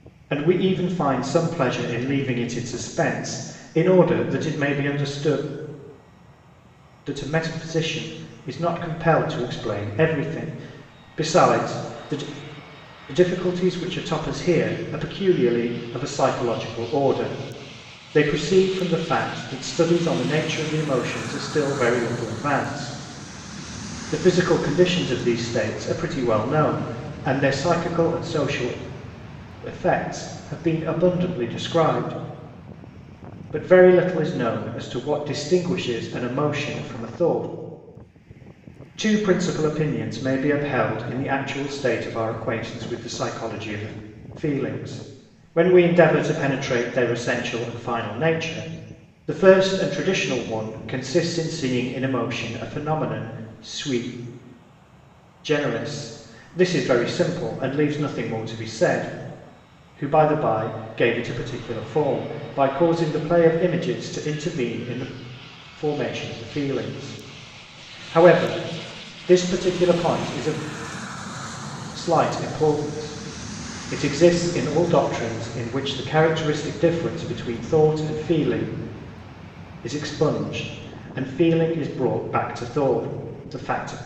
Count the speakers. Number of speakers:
1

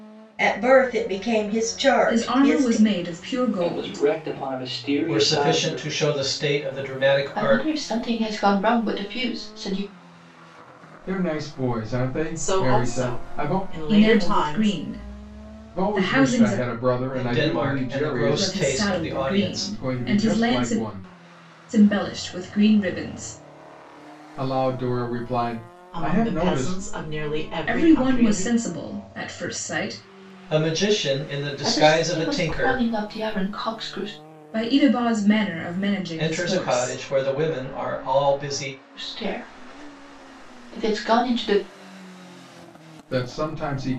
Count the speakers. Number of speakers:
7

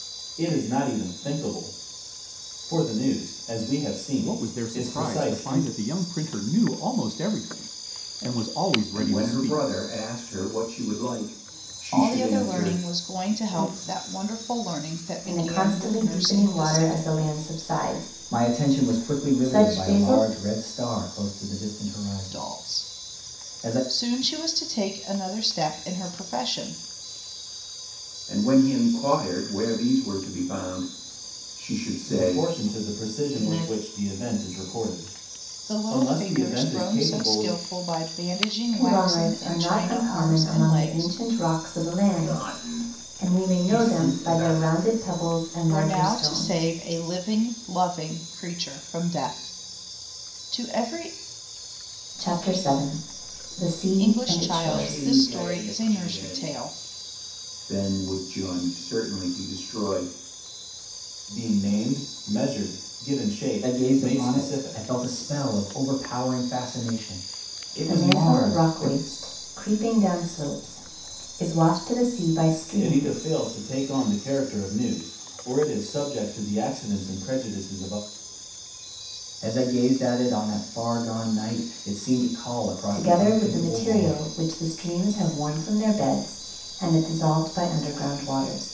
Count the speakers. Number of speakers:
6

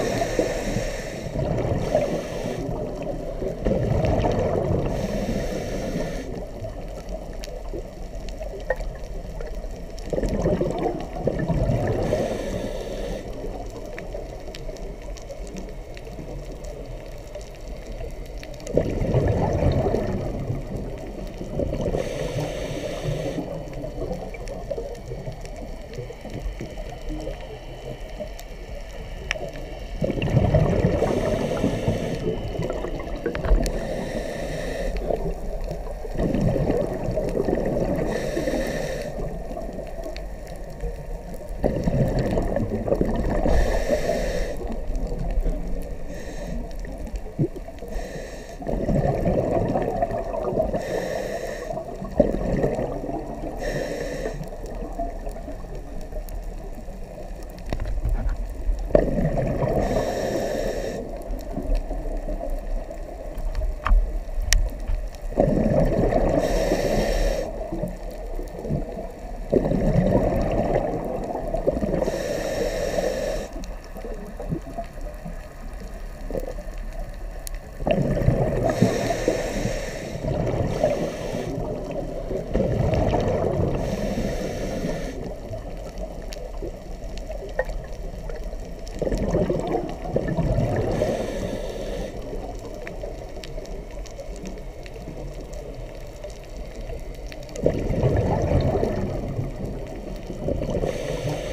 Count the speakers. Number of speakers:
0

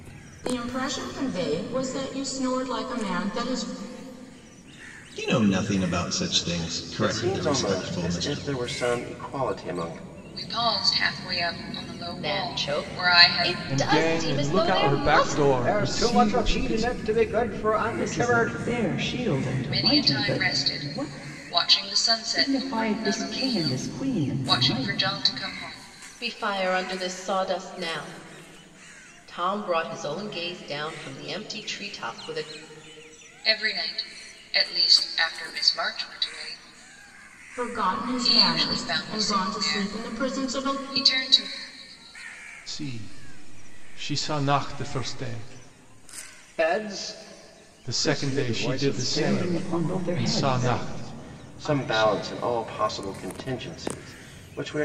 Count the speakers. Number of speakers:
8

